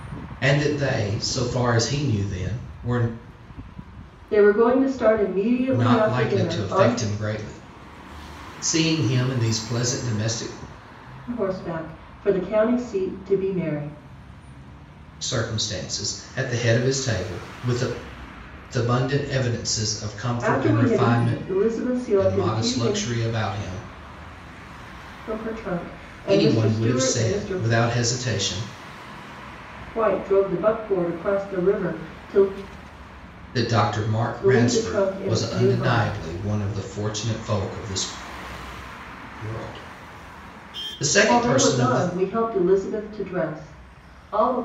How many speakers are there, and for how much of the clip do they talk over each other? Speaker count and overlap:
two, about 16%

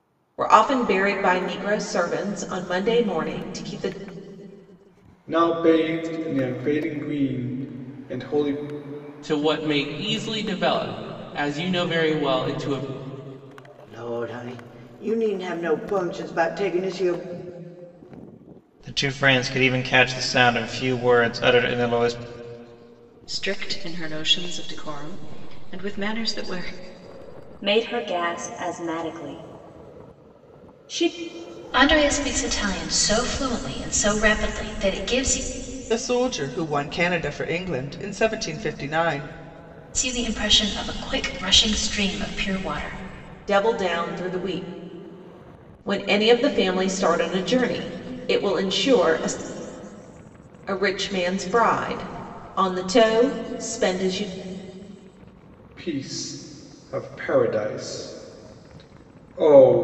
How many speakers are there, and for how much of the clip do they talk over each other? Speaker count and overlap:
nine, no overlap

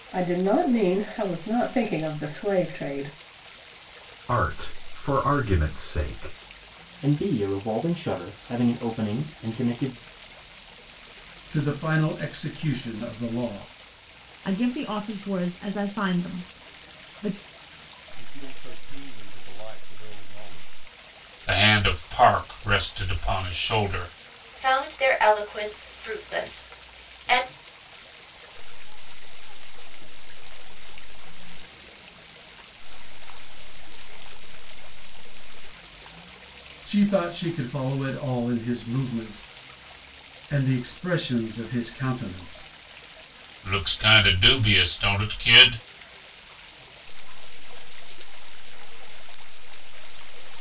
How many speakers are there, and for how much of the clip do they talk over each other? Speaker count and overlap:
nine, no overlap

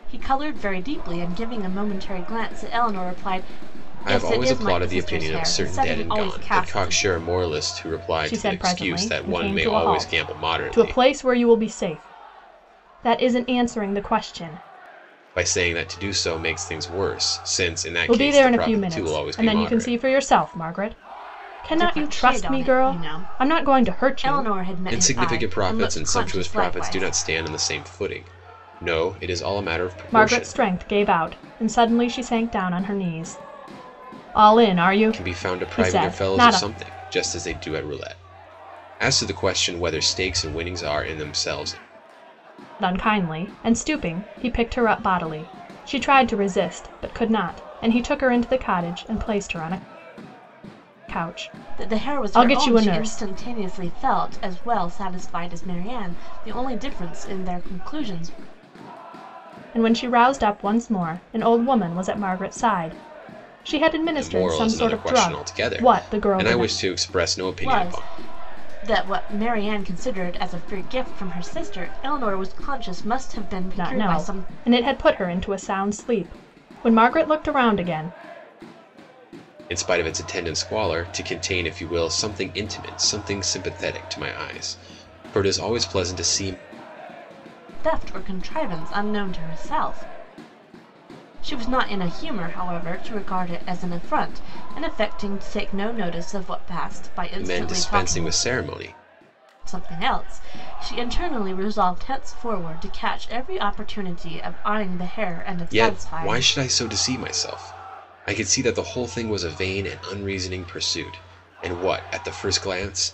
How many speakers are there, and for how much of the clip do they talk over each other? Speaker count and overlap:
three, about 20%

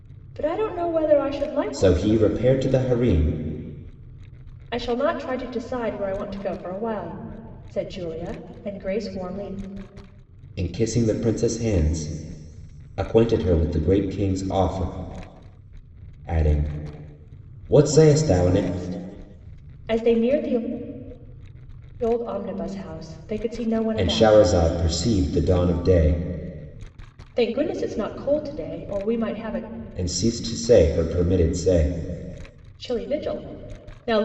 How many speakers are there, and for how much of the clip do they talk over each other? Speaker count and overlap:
two, about 4%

